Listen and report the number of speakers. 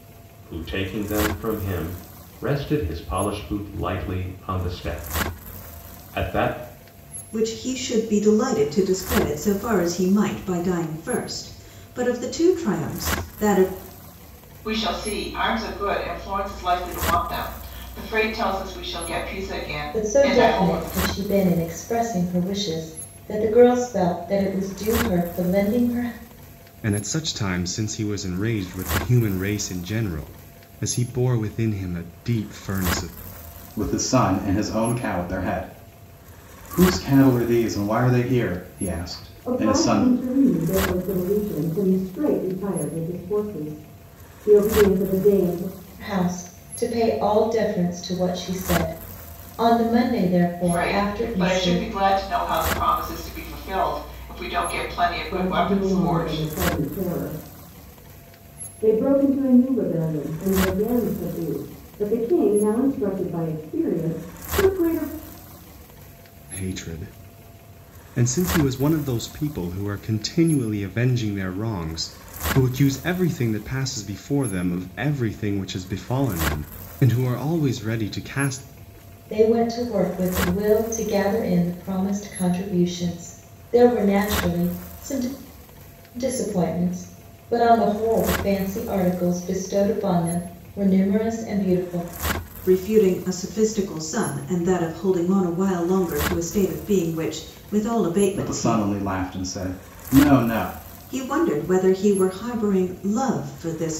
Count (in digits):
7